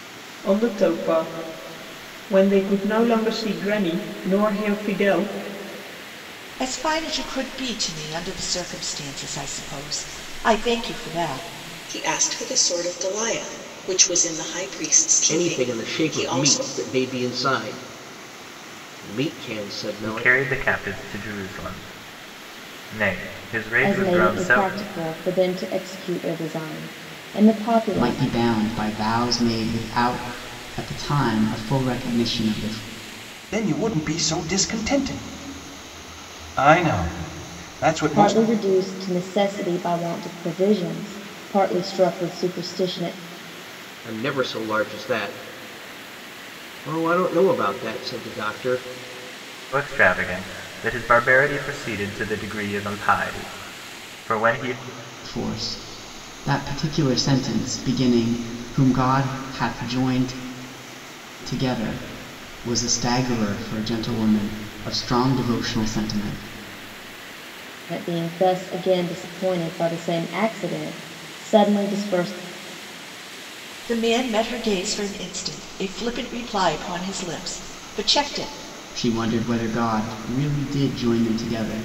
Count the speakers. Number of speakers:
8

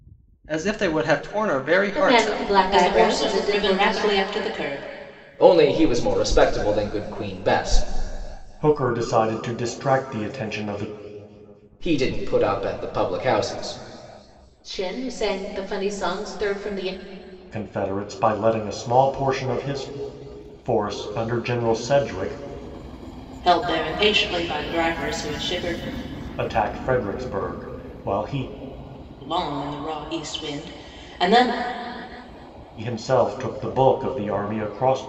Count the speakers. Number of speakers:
5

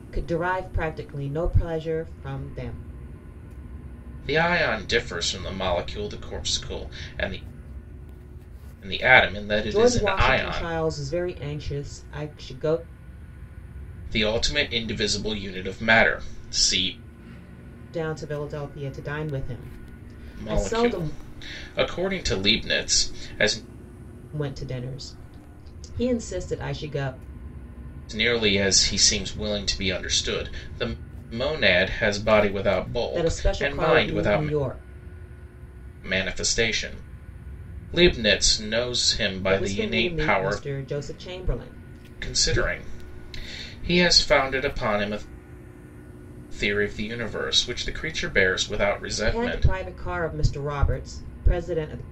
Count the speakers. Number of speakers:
2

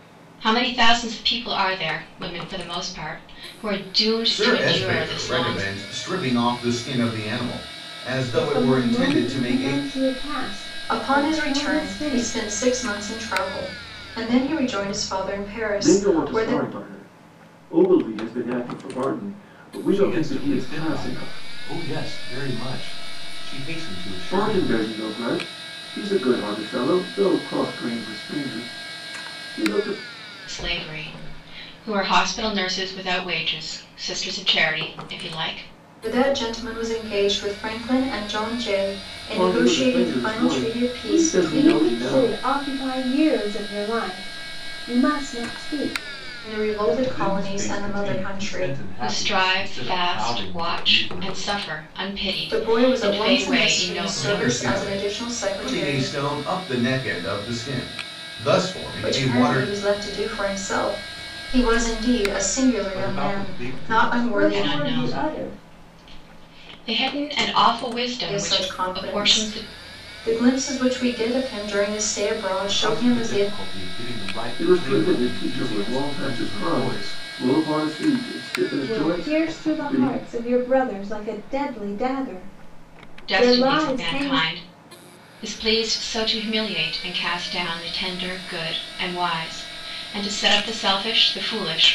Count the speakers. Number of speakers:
6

